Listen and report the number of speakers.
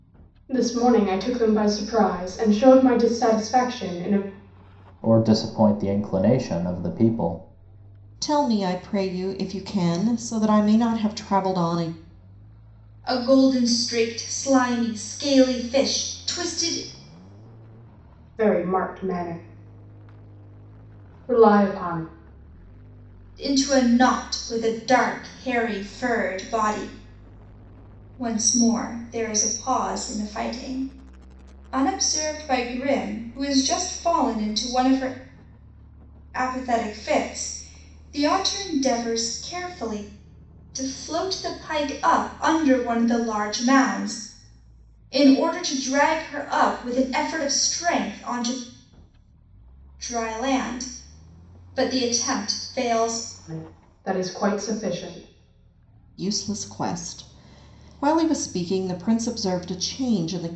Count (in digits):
4